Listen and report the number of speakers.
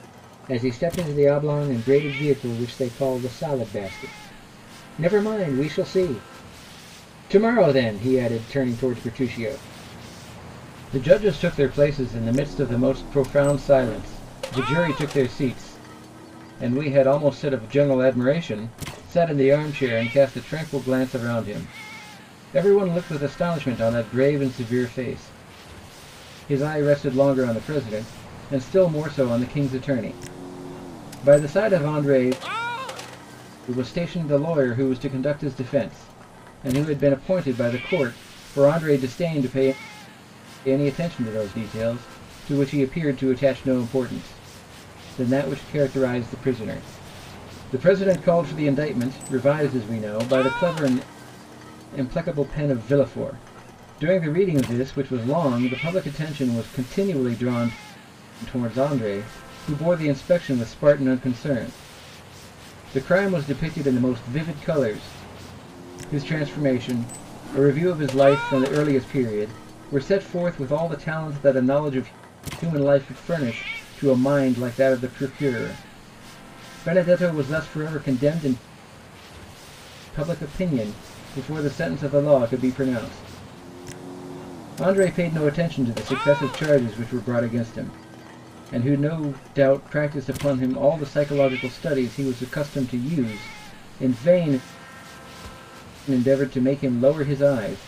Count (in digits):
1